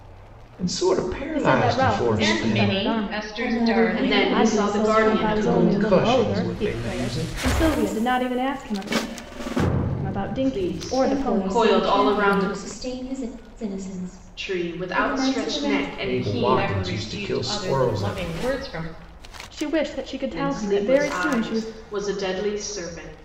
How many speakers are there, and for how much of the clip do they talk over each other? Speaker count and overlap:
five, about 61%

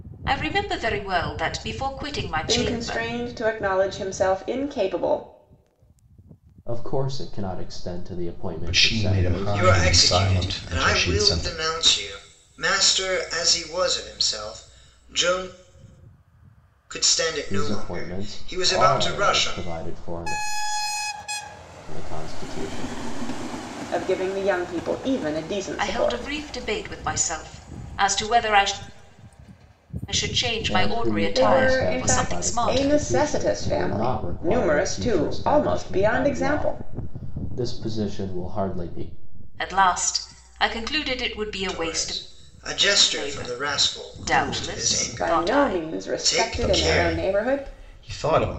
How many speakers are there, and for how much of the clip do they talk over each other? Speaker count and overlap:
five, about 36%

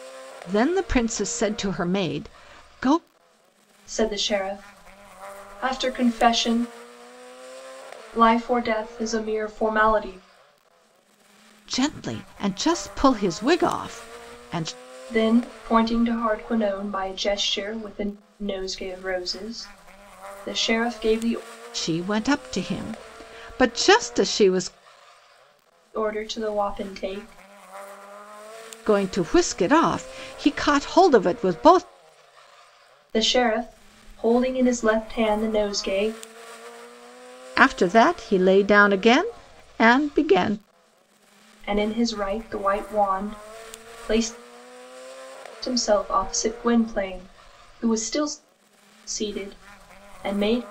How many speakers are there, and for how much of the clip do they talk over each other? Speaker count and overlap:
two, no overlap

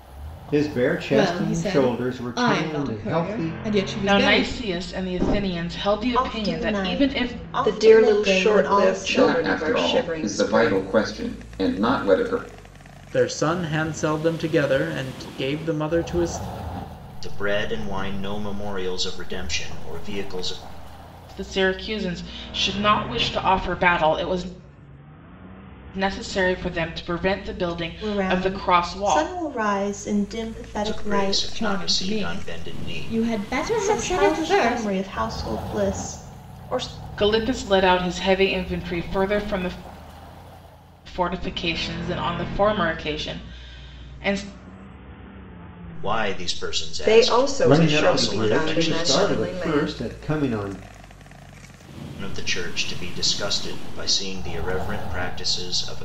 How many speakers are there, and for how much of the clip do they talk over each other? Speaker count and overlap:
eight, about 27%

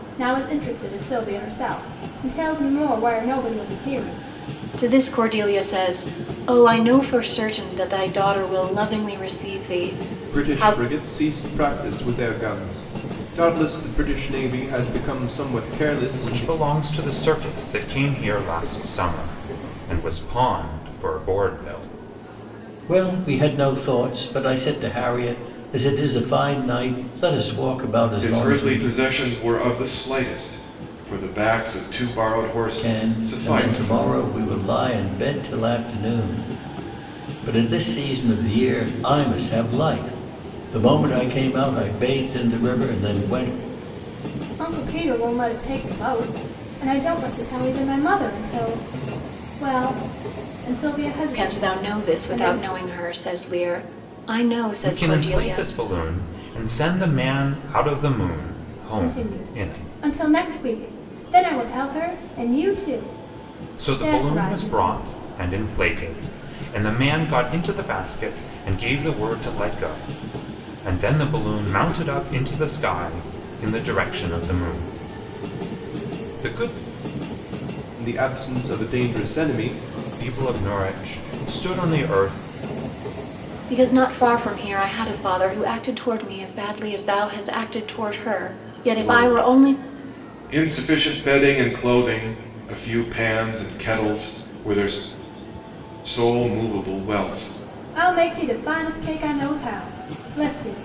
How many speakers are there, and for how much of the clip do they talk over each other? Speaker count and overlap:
six, about 8%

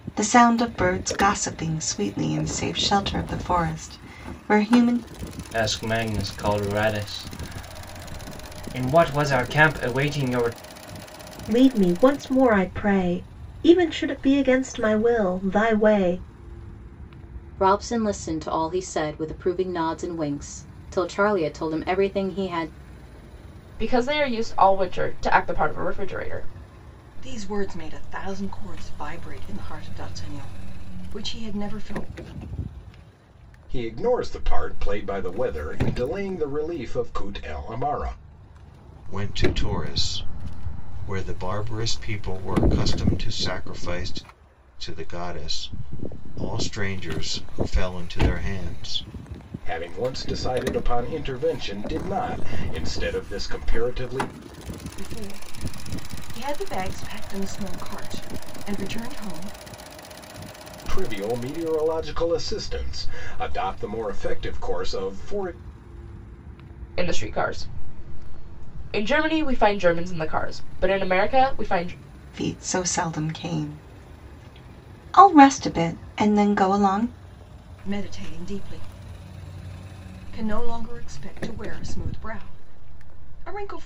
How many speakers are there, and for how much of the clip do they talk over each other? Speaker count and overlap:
eight, no overlap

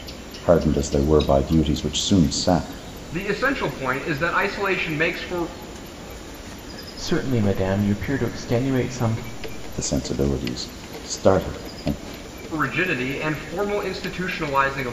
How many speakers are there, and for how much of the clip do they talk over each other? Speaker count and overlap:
three, no overlap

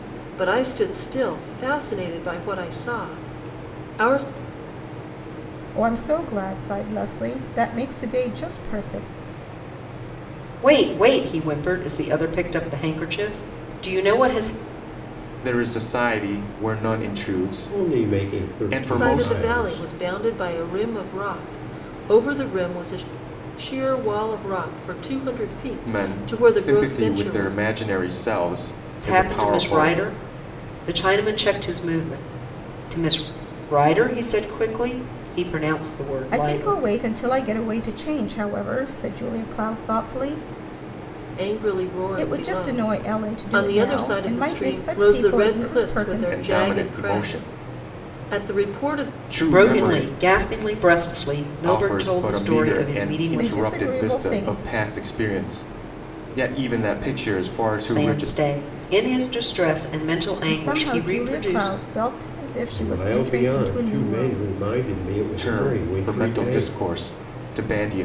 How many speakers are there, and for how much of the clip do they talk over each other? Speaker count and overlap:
five, about 31%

